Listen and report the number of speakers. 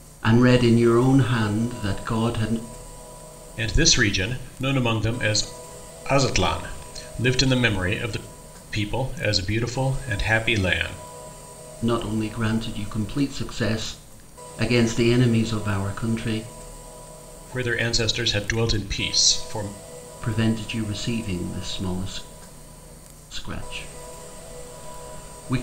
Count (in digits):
2